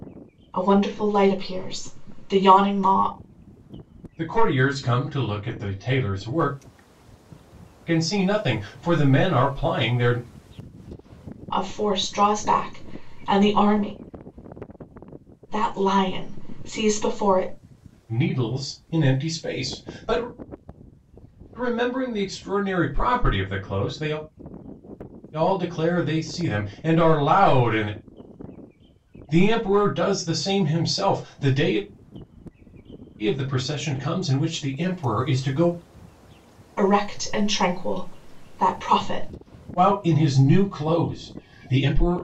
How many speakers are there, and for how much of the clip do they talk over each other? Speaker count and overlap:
two, no overlap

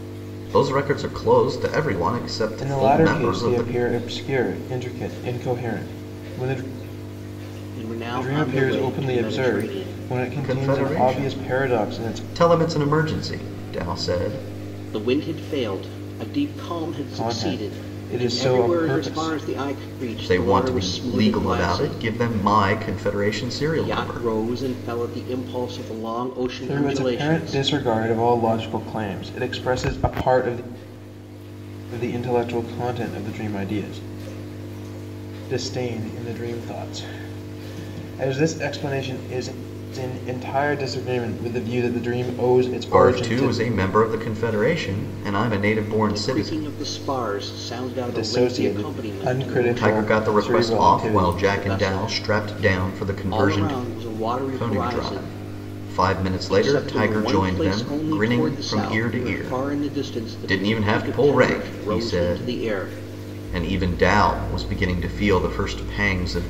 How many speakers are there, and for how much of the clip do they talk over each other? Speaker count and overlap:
three, about 37%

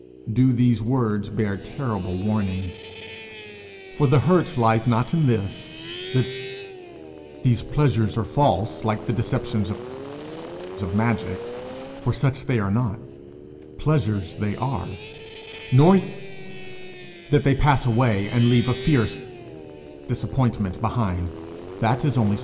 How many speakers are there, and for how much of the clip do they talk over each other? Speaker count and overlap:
one, no overlap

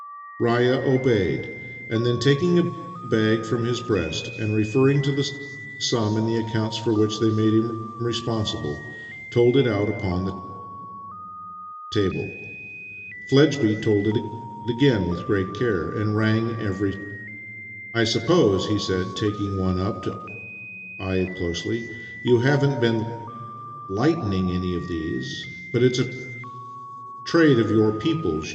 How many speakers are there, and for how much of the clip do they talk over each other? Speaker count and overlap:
one, no overlap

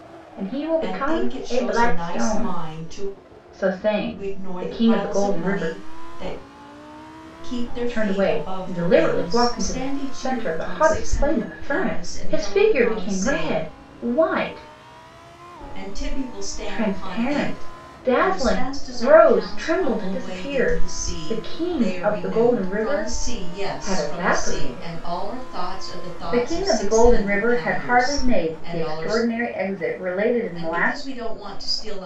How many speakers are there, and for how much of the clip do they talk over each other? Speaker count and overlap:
two, about 60%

